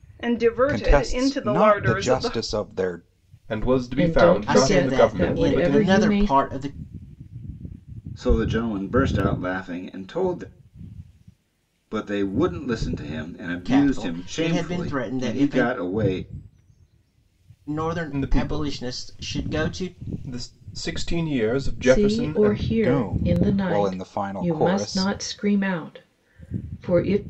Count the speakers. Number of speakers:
6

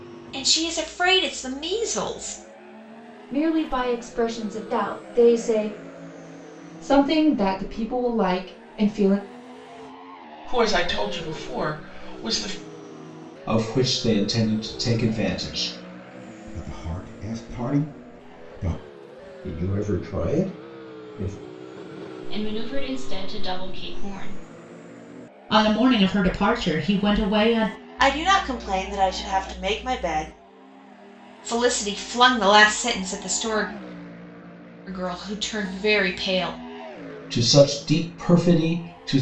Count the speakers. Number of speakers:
10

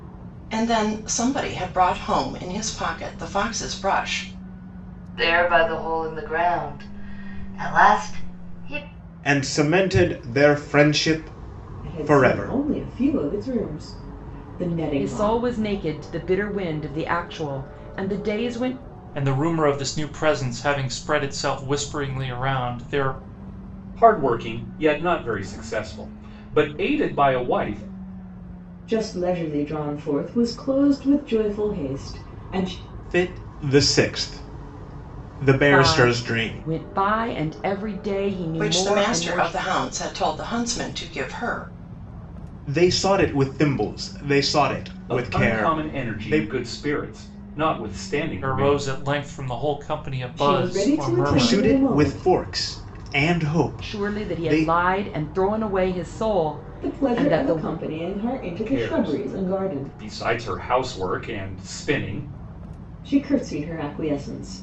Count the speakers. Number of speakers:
7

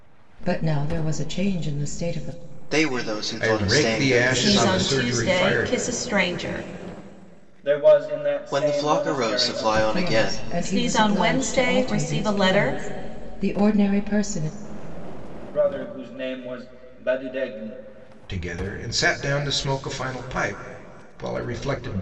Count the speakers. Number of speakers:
5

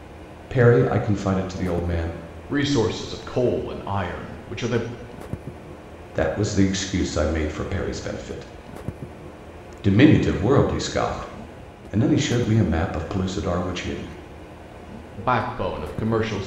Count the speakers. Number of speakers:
2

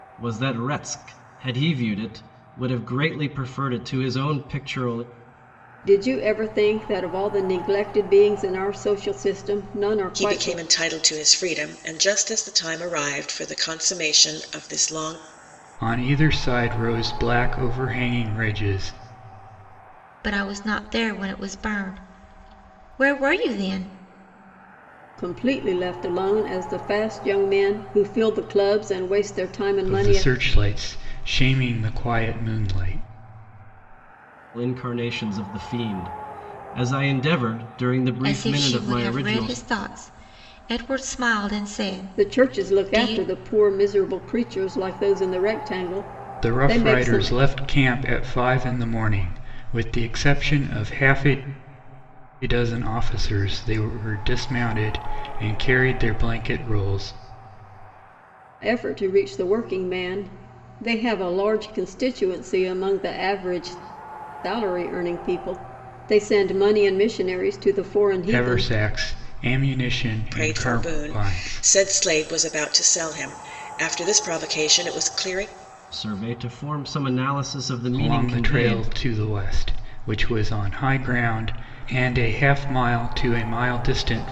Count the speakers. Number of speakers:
5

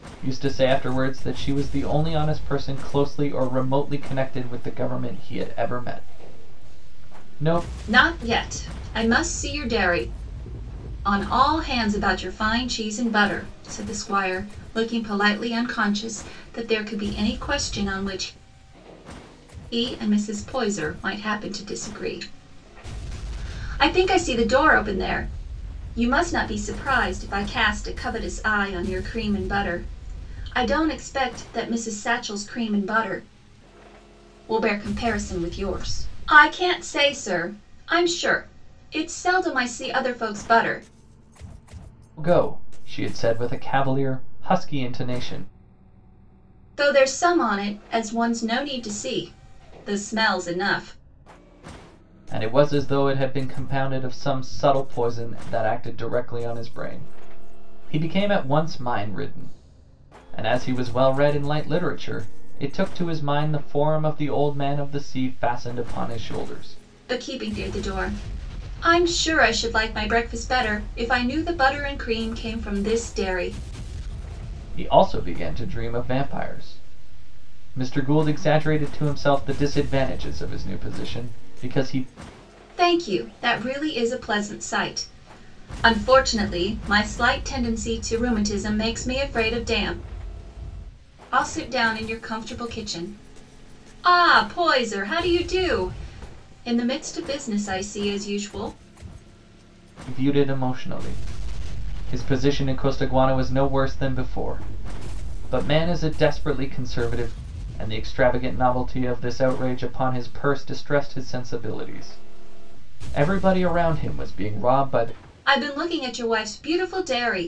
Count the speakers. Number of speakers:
2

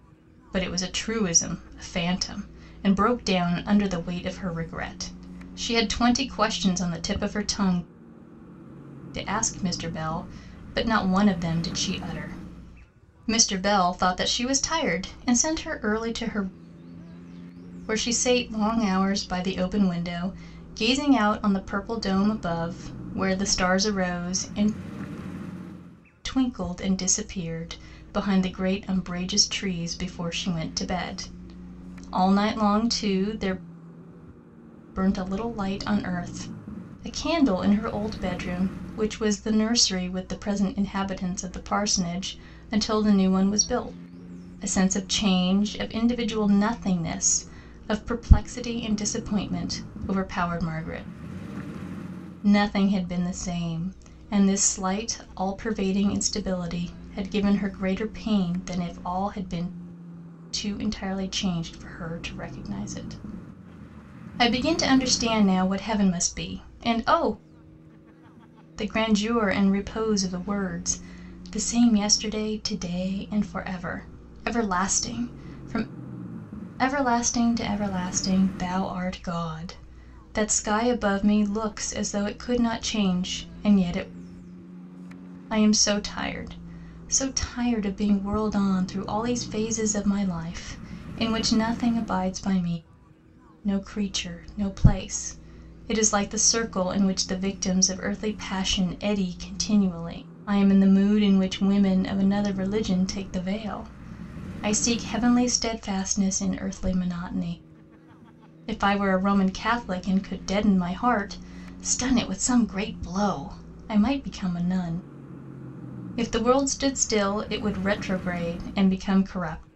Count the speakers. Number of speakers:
1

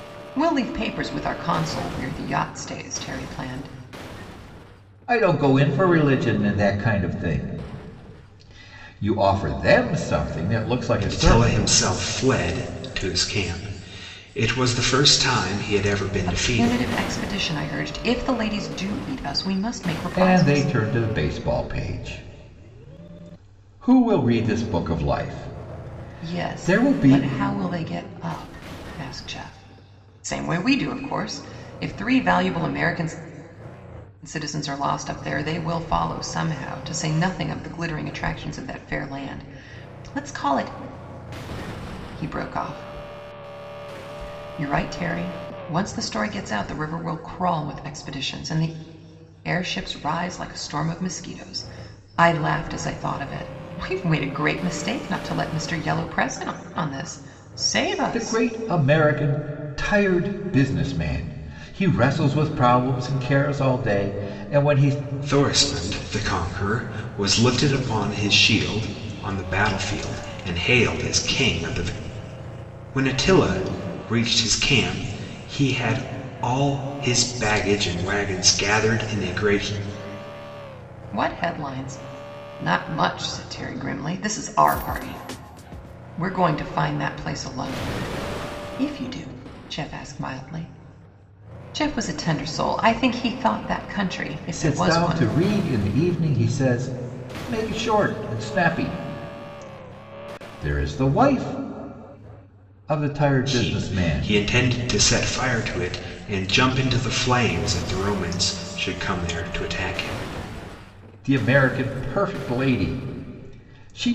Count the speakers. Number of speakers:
3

